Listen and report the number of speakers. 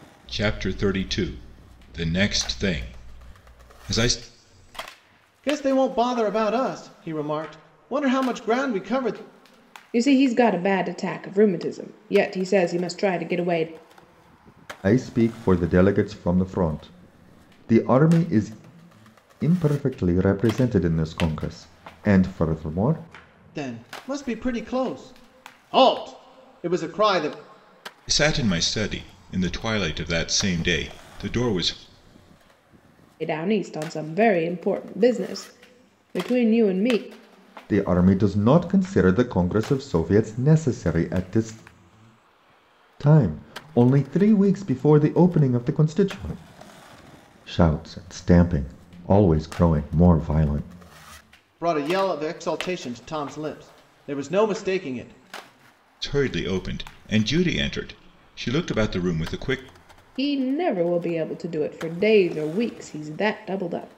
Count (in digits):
4